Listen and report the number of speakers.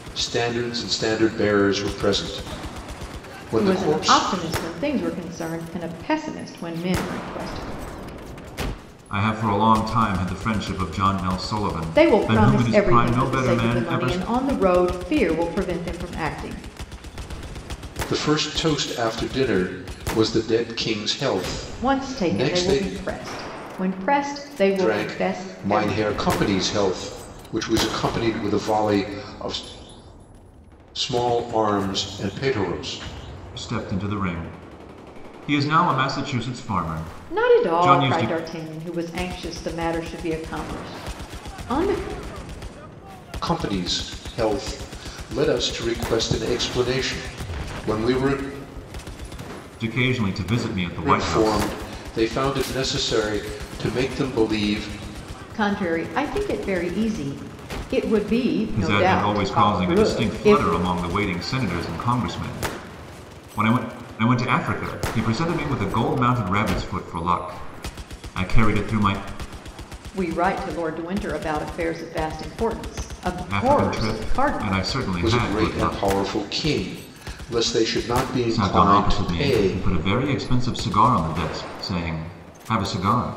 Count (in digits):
3